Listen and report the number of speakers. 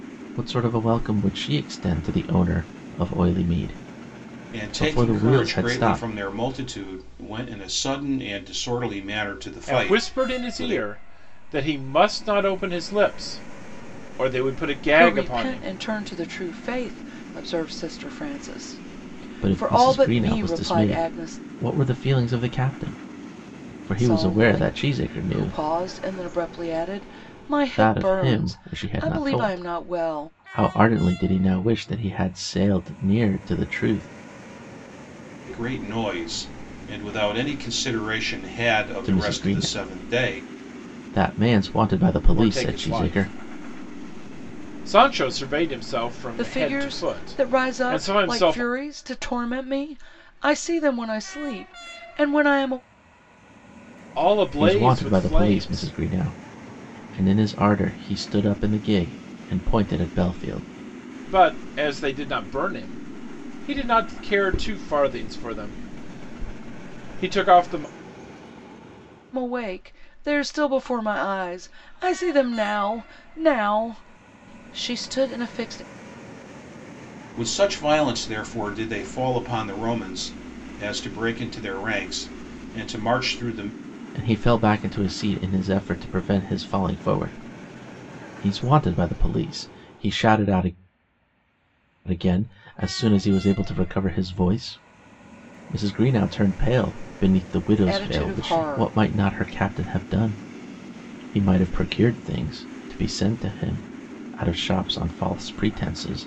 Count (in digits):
4